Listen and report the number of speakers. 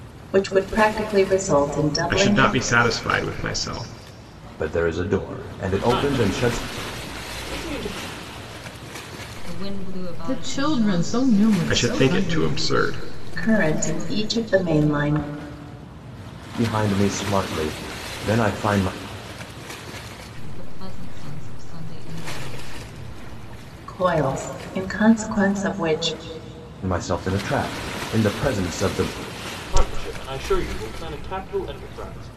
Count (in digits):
6